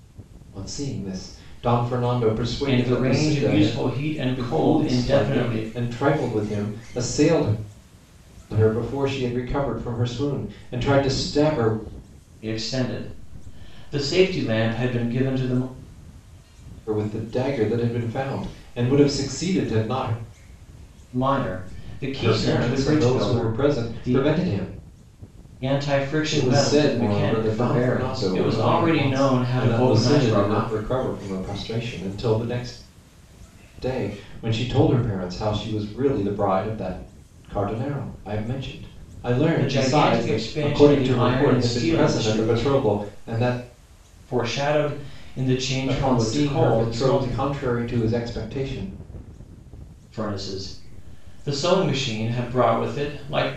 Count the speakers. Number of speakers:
2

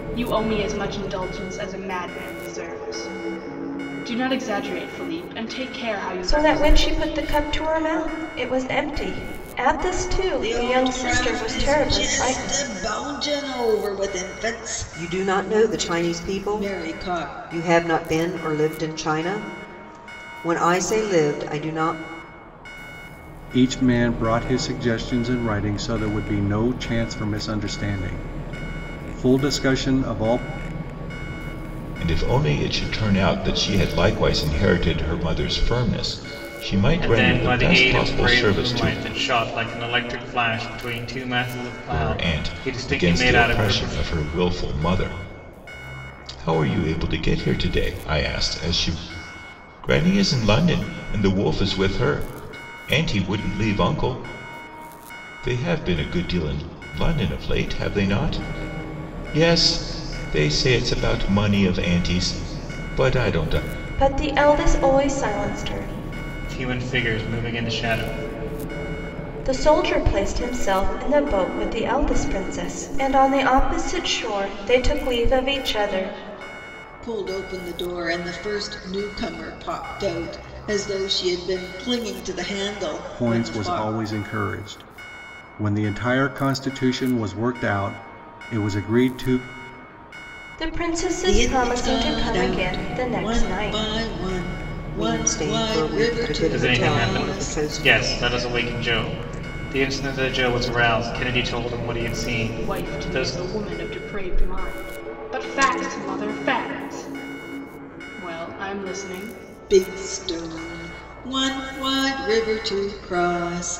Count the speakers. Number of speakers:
7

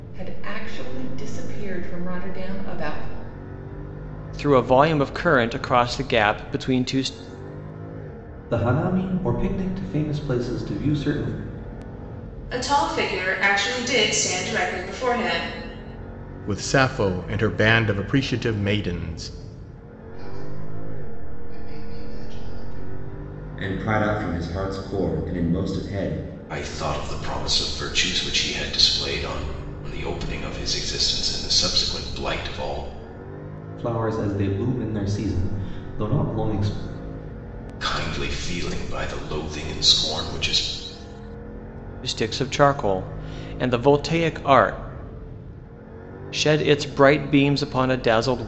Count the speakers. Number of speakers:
8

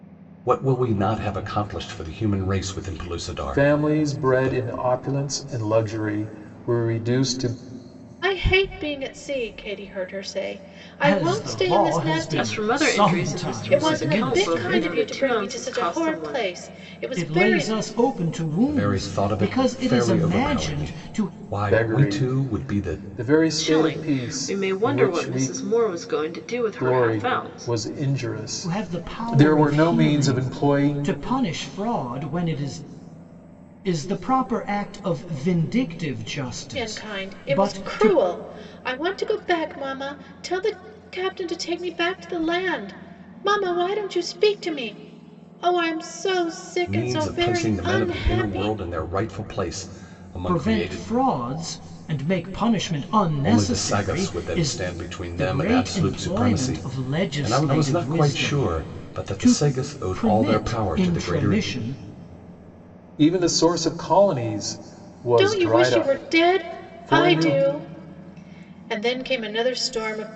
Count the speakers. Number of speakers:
5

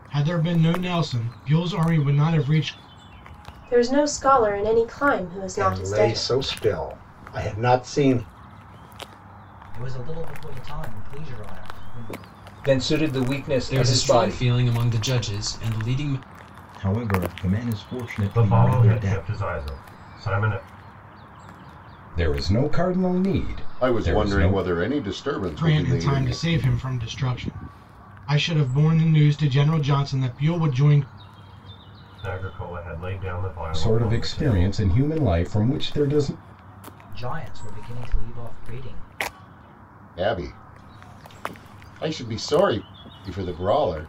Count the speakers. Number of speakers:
10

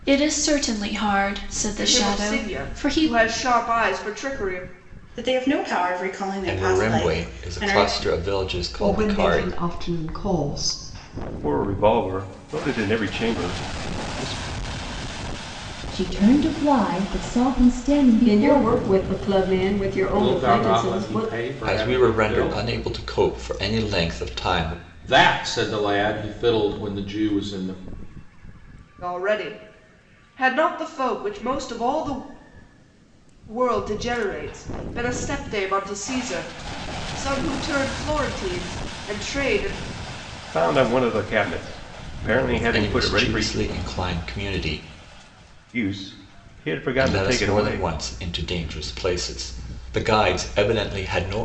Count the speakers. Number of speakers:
9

